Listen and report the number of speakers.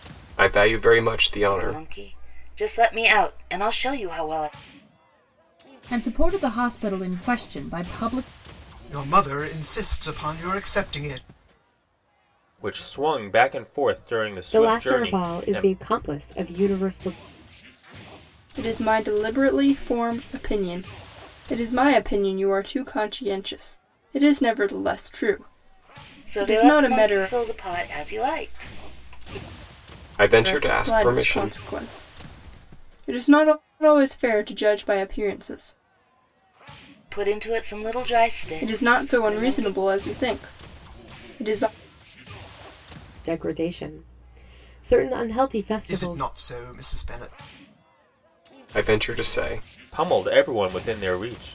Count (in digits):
7